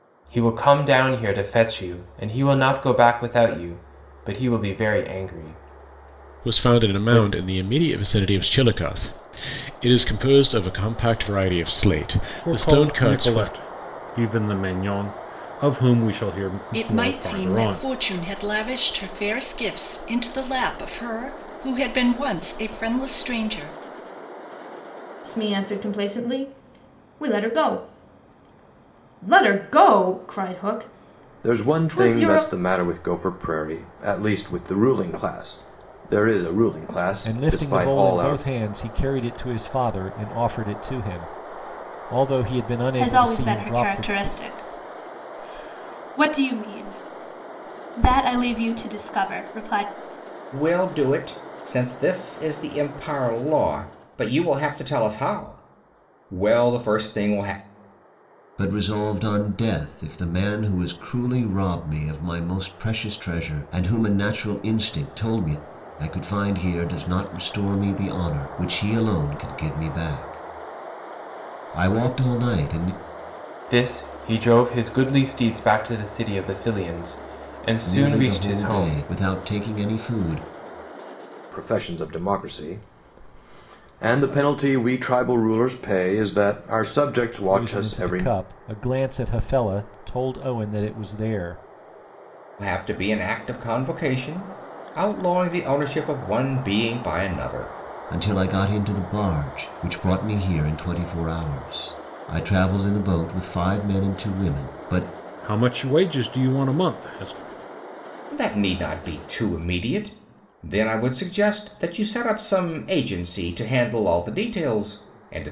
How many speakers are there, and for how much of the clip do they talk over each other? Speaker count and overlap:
ten, about 8%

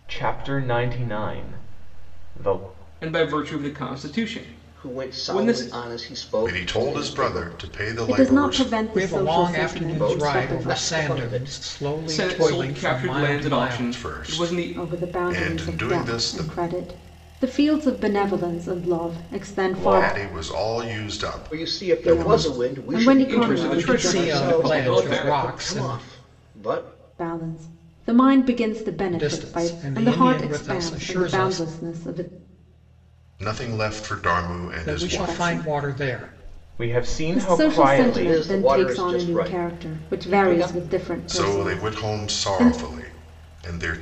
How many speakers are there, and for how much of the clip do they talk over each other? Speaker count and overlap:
six, about 56%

